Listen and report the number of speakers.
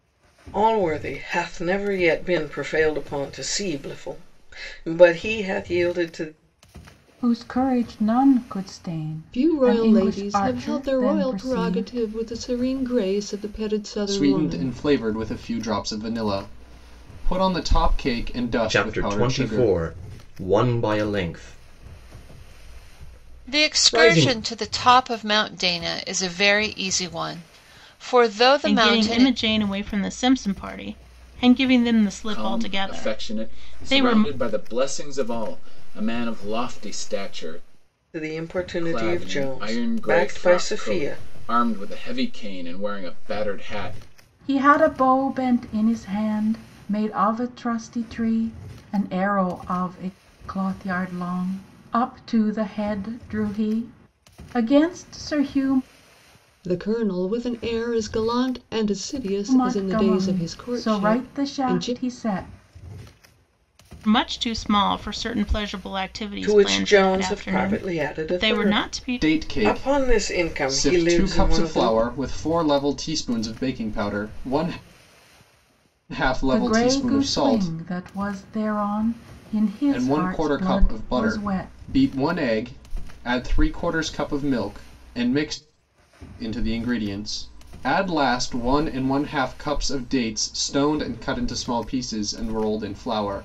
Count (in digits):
8